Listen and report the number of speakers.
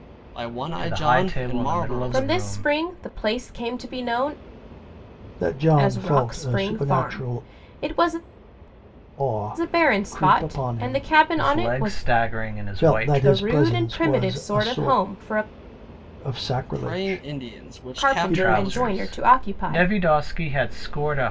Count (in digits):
4